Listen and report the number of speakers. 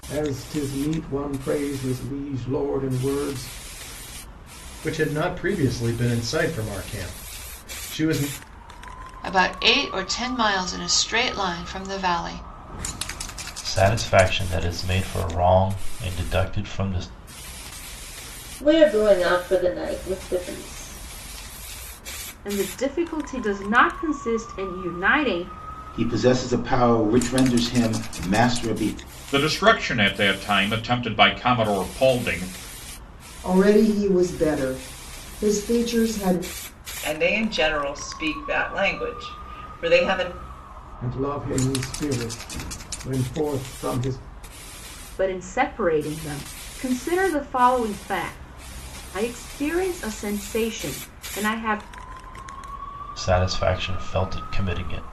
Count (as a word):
ten